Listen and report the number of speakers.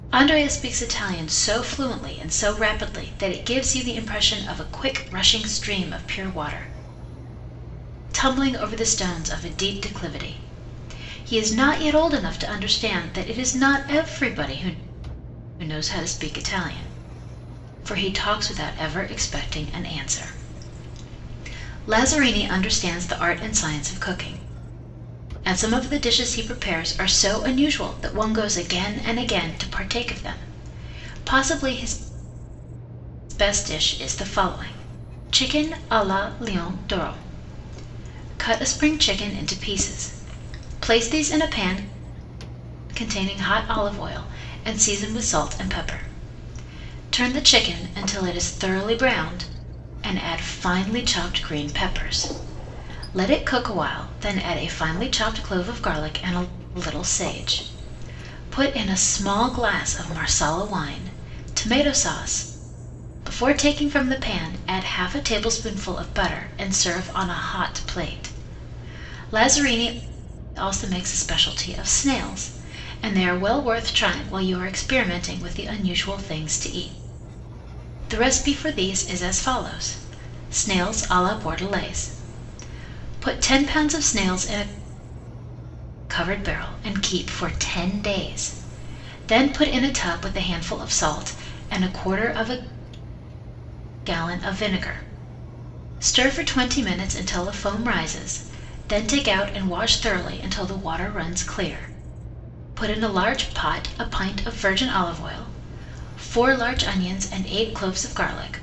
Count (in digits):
1